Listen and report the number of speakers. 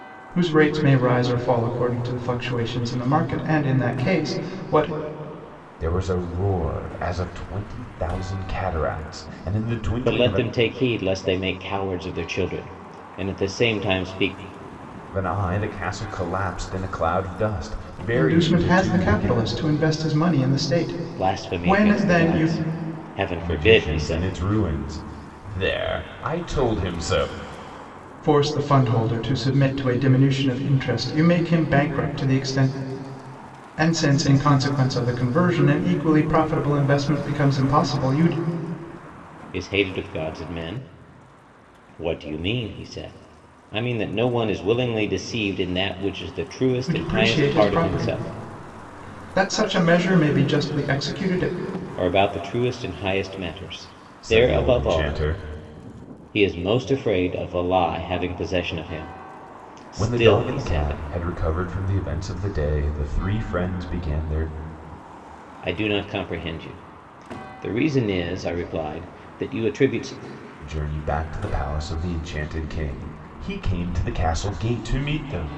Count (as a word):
three